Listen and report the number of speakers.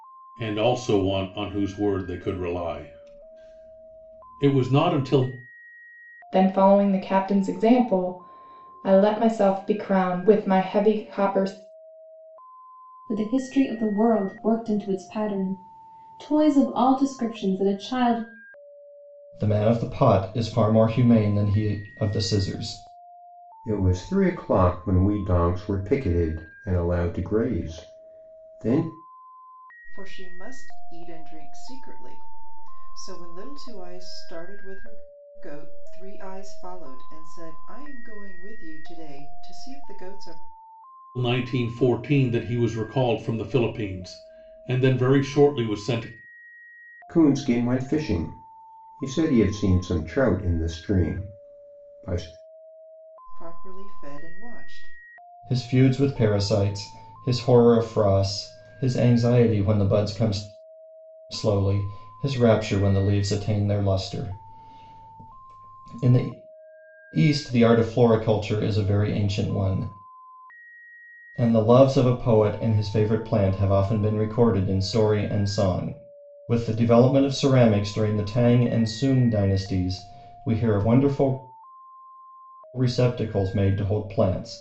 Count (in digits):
6